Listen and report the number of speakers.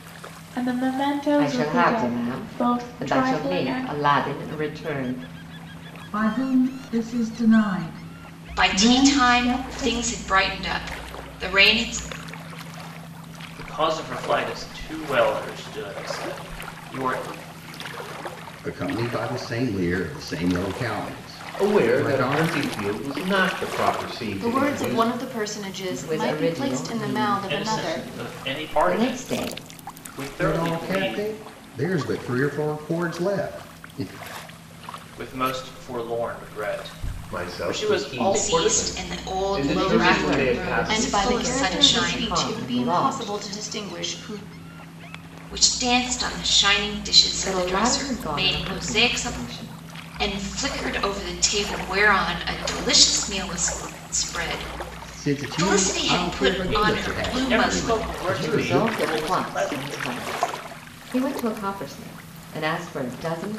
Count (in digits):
8